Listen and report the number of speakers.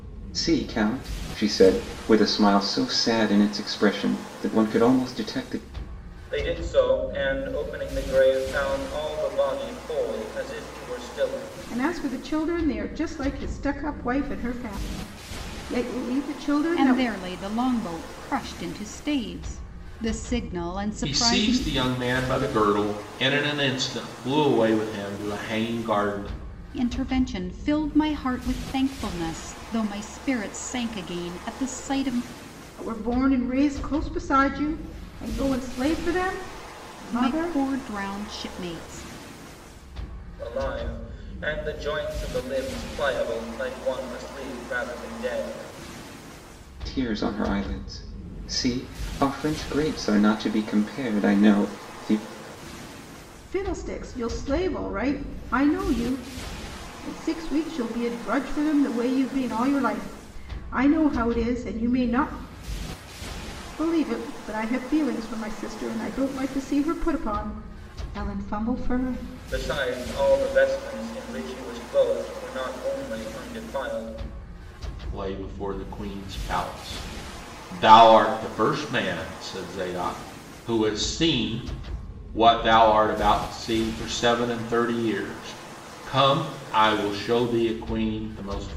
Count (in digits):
5